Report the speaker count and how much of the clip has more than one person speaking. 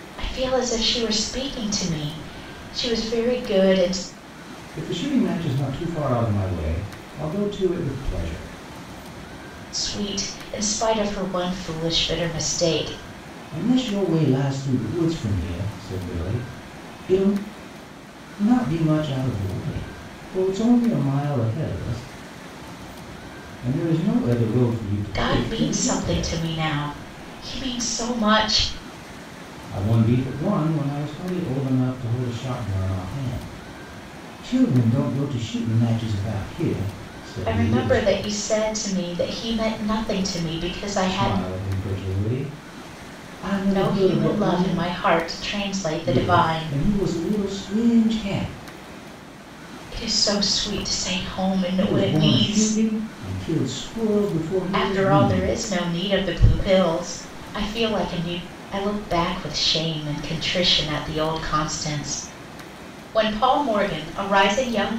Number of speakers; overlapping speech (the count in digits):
2, about 9%